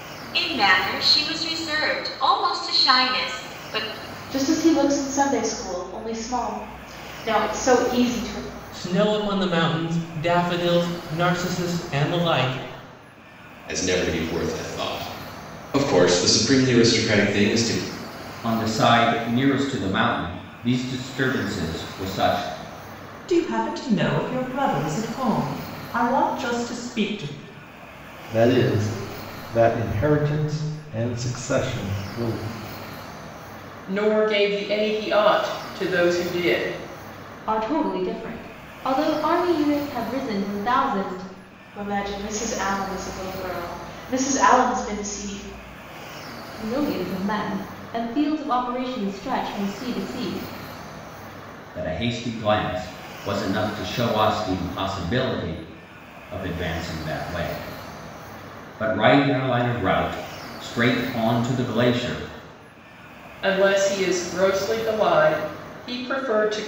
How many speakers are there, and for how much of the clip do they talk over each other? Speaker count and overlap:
nine, no overlap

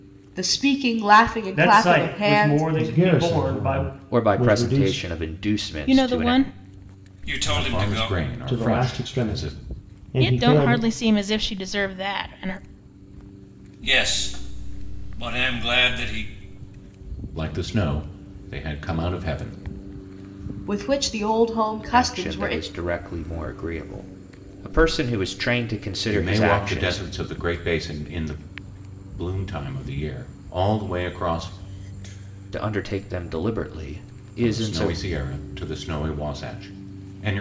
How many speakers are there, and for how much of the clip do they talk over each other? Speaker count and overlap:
seven, about 24%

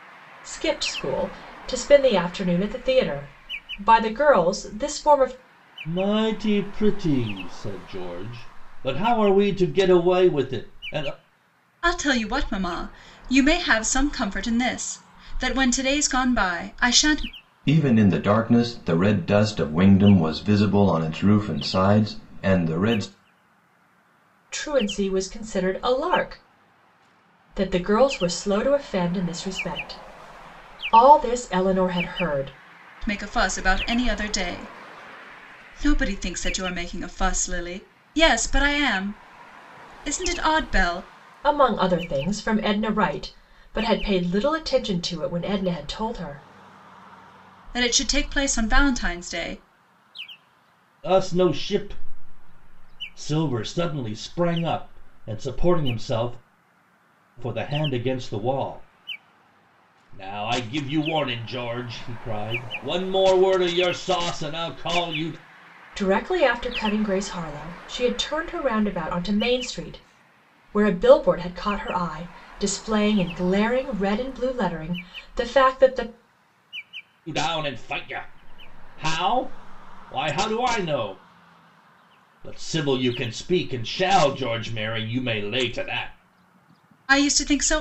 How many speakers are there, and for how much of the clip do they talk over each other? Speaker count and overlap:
four, no overlap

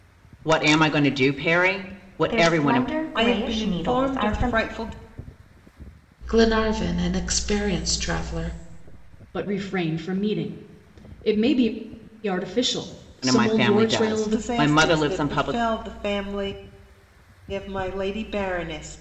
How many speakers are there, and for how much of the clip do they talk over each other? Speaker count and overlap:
five, about 24%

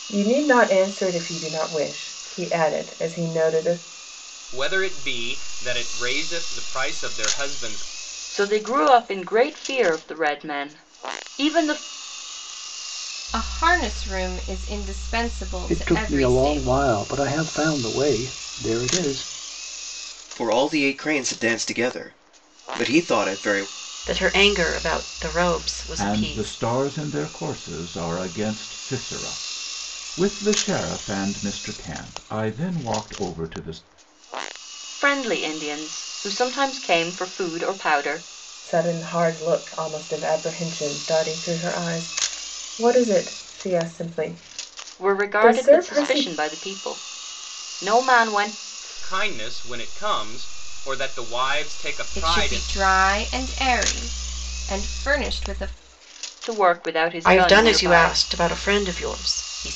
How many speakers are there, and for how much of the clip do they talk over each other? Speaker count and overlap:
eight, about 8%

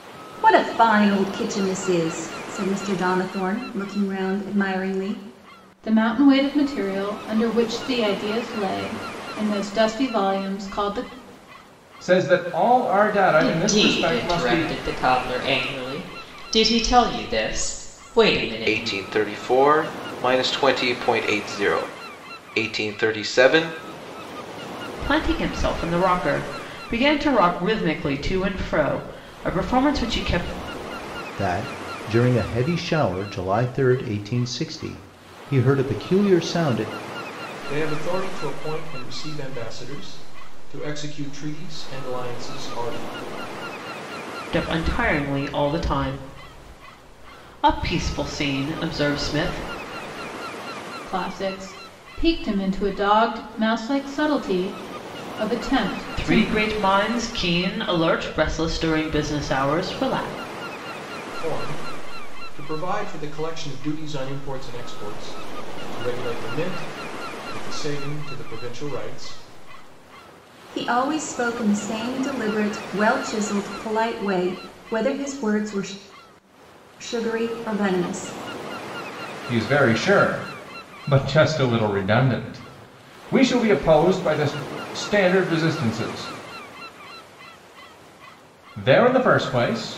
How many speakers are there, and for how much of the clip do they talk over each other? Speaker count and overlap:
eight, about 2%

